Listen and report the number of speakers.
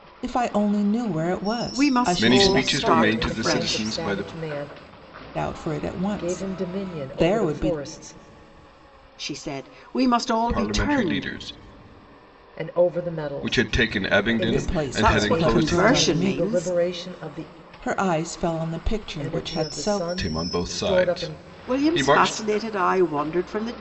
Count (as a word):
four